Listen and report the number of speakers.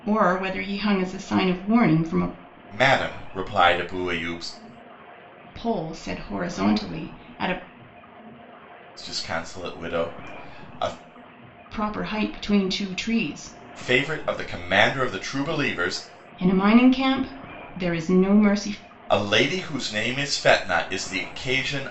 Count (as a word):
two